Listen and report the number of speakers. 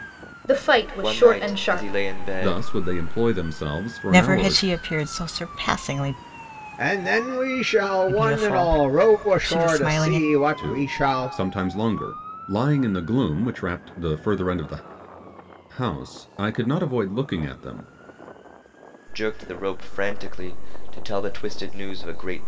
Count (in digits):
5